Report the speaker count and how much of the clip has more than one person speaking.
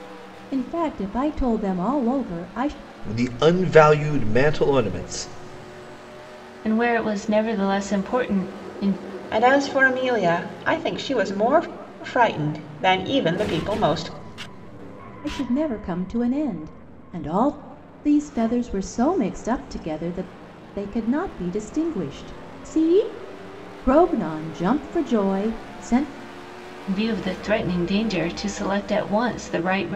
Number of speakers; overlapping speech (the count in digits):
4, no overlap